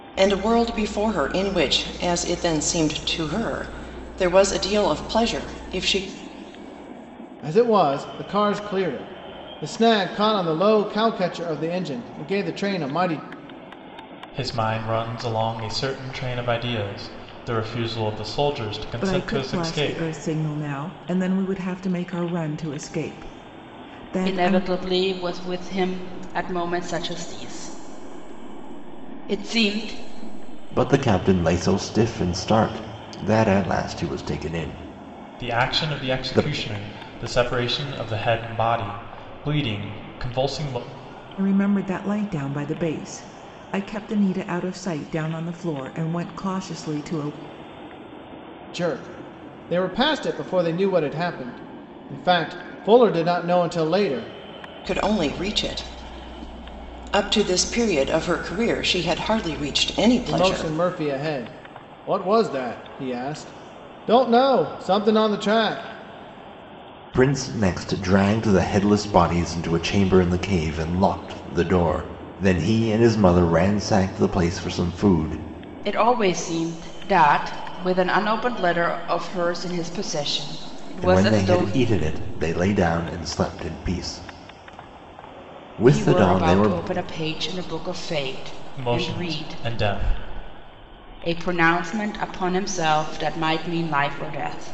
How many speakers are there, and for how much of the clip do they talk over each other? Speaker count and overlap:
6, about 6%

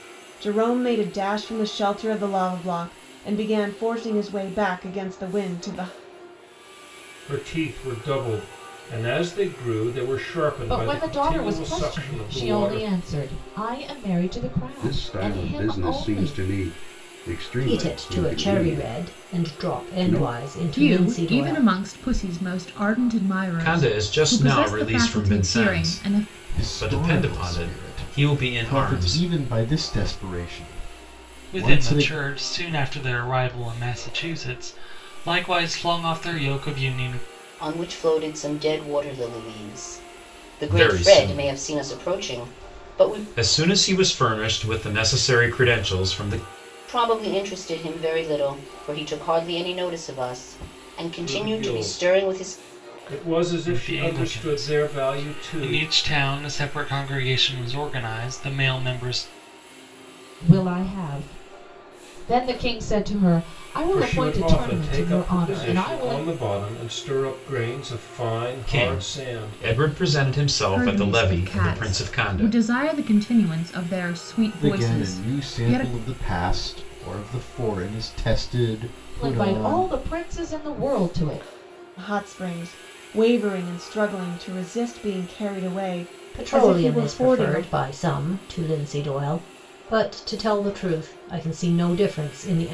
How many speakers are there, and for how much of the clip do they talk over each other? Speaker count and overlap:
10, about 31%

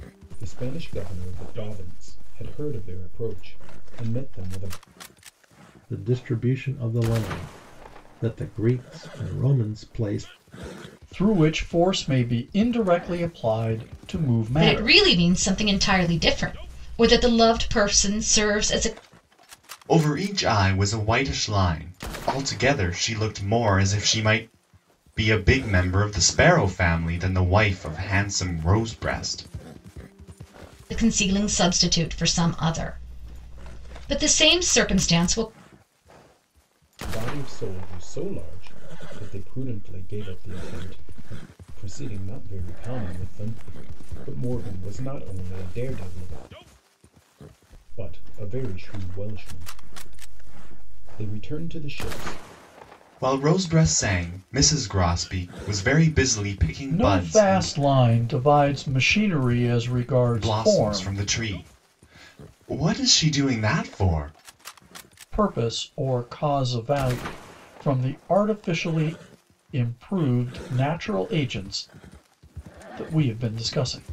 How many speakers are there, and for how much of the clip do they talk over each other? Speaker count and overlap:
5, about 3%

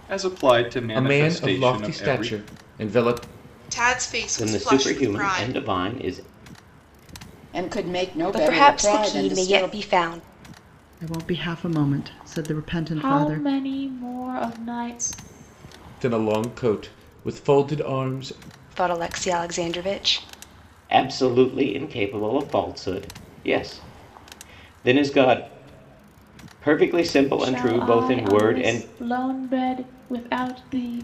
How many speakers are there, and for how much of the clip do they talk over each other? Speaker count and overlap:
8, about 20%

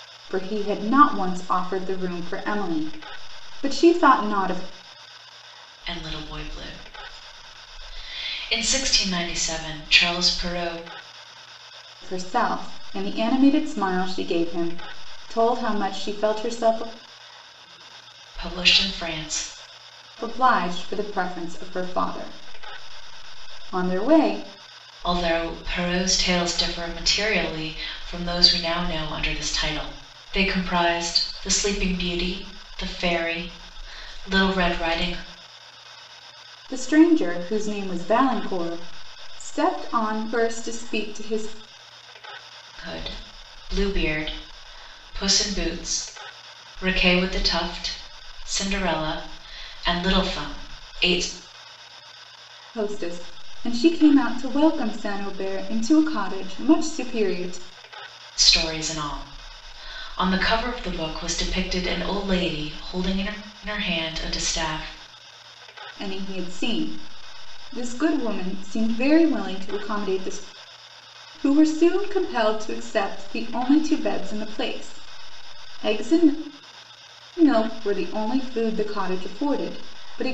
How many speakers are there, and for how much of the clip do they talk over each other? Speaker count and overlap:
2, no overlap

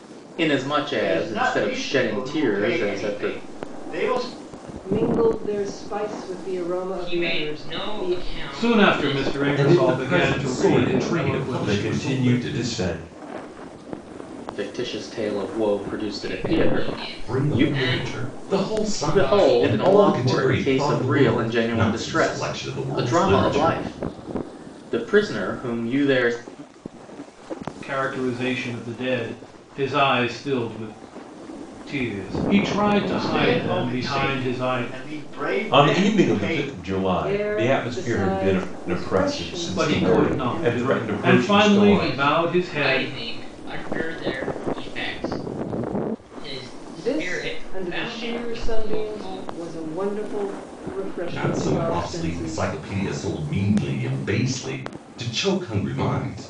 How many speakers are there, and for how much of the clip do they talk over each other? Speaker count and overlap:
7, about 48%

